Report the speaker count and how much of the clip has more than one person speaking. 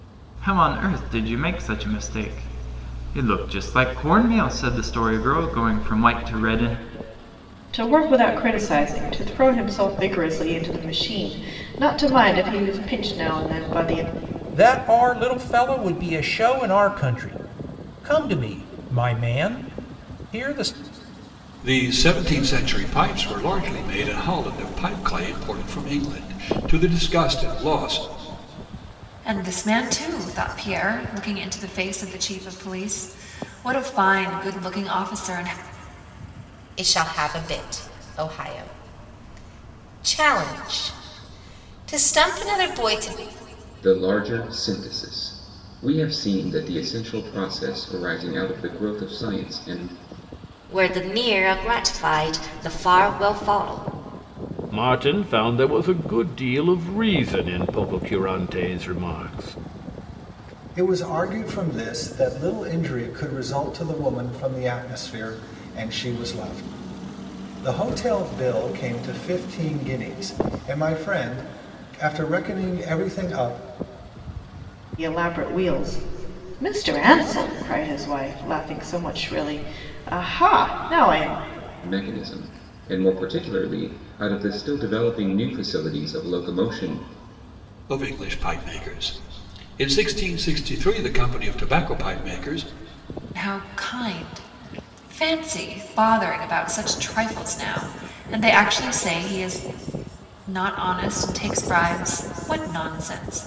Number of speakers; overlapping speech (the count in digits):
10, no overlap